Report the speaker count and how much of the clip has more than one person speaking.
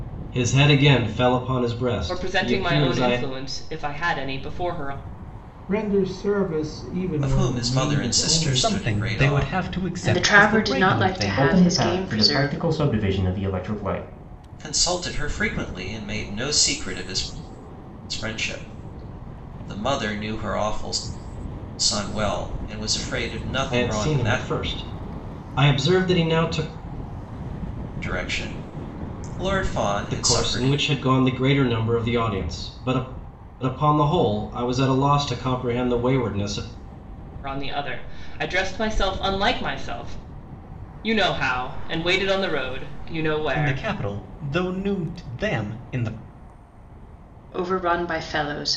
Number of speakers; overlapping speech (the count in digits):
7, about 17%